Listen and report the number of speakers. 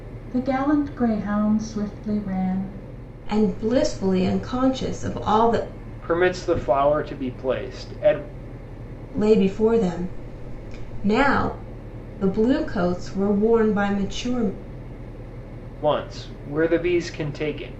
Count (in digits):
3